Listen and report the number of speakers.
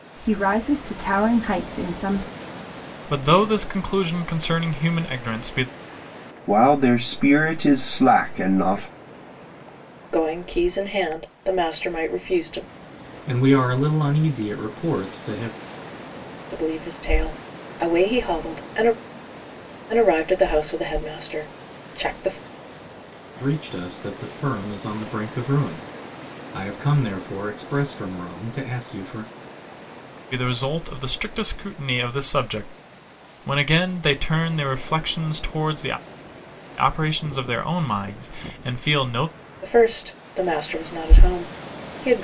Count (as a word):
five